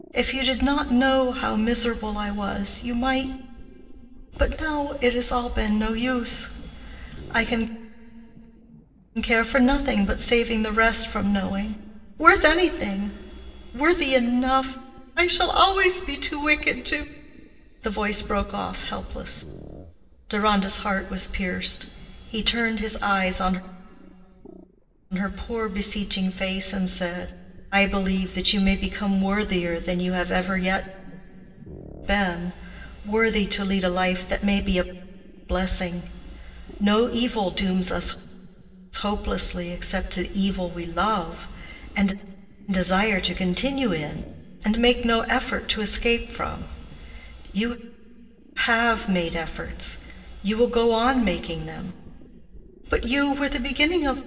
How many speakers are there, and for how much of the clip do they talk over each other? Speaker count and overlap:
1, no overlap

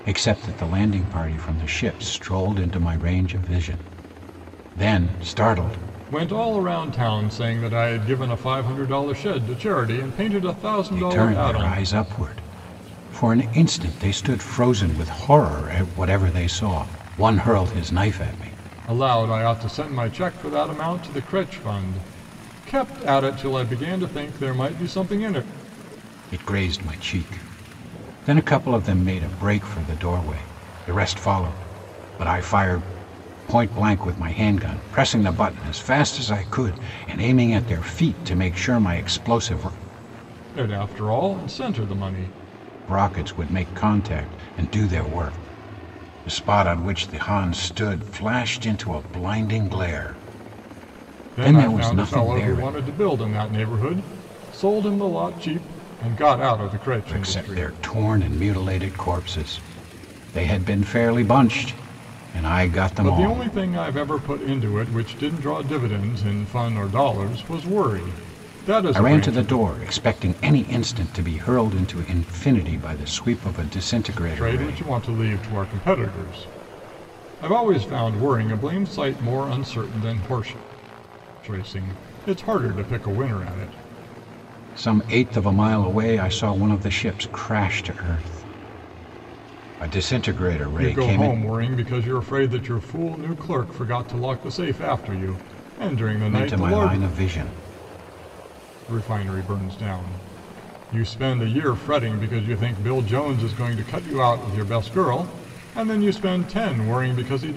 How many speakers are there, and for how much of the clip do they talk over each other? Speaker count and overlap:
2, about 6%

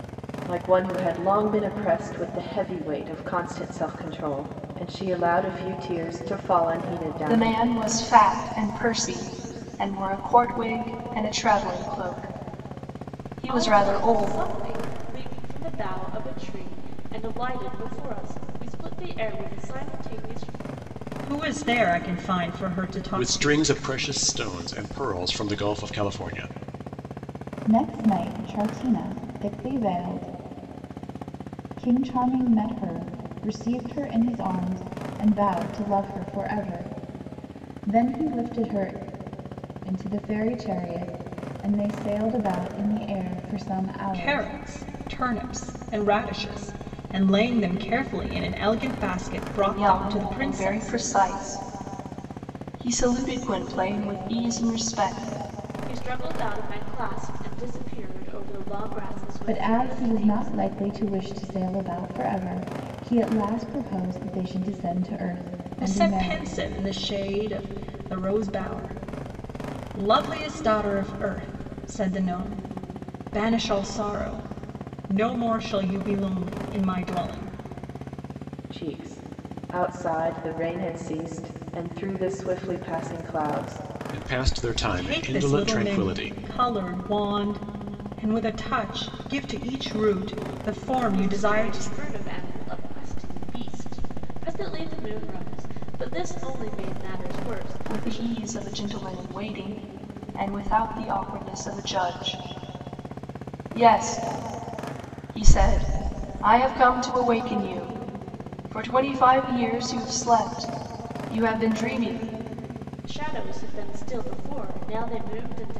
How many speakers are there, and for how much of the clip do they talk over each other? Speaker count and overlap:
6, about 7%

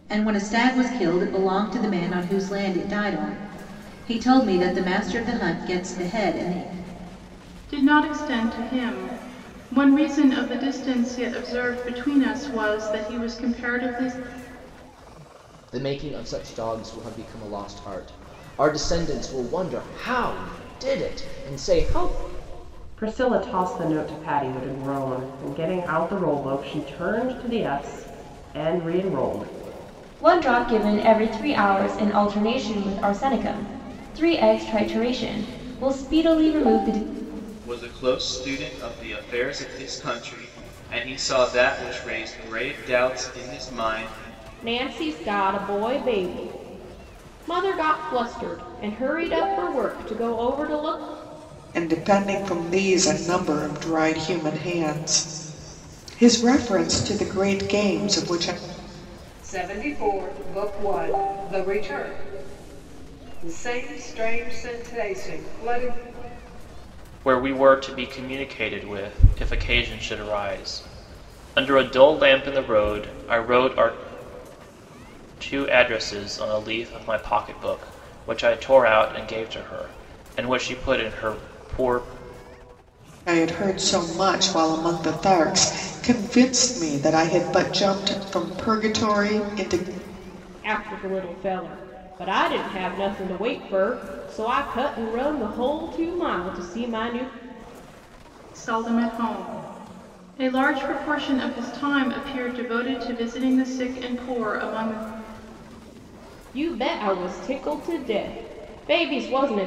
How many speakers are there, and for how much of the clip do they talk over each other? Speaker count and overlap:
10, no overlap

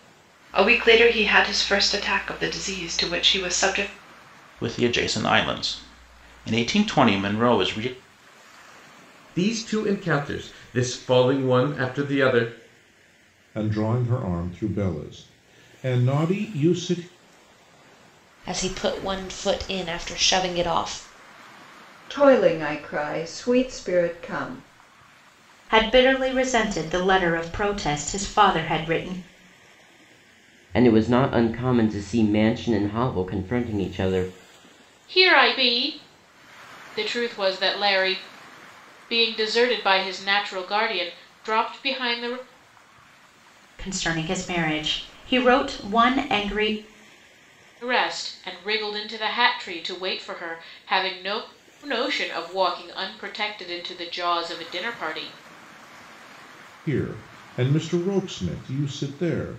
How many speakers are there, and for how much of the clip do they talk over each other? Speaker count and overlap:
9, no overlap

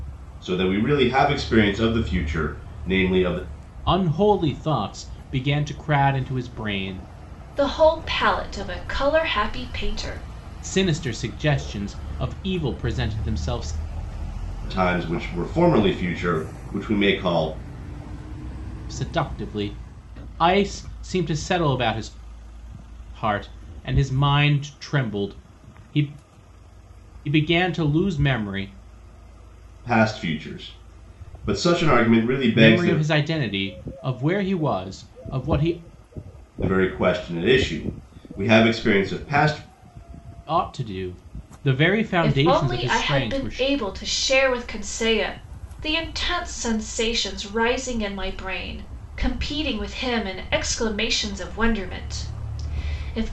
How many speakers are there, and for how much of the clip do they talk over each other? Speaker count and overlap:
3, about 4%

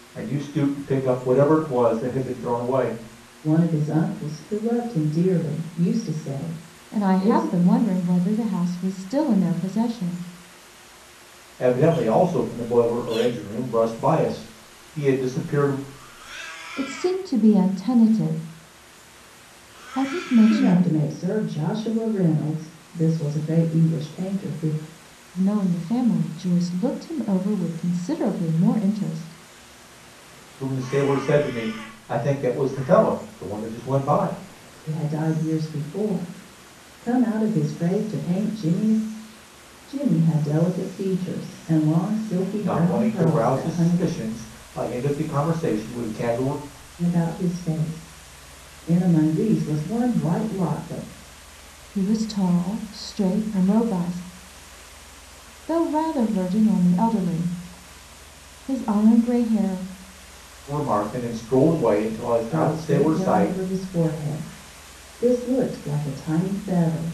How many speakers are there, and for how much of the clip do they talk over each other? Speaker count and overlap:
3, about 5%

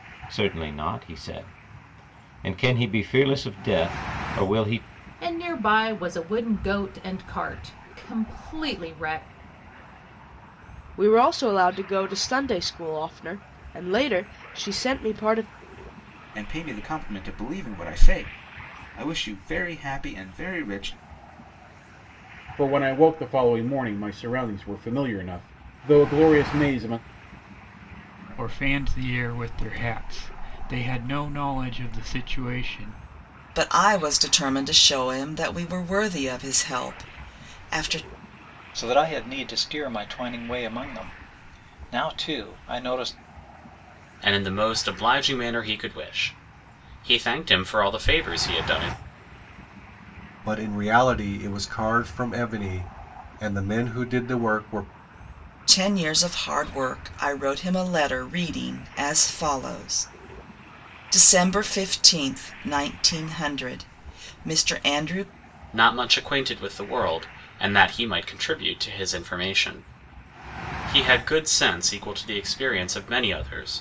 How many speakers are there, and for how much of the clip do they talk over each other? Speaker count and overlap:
10, no overlap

